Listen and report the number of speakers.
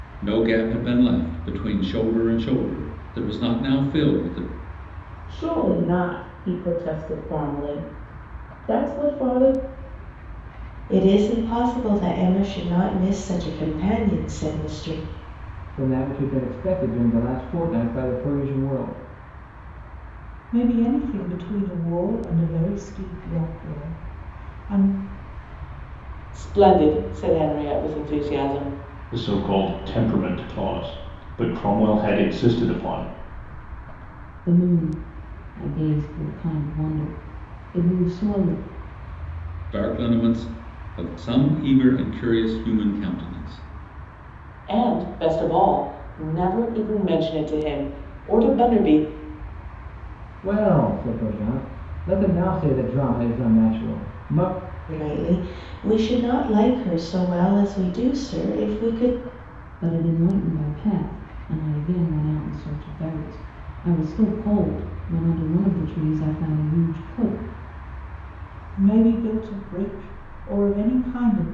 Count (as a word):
eight